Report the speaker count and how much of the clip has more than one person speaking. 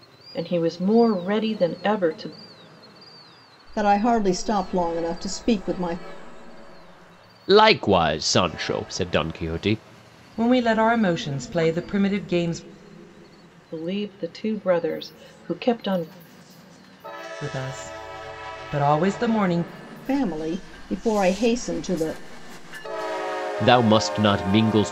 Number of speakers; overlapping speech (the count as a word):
four, no overlap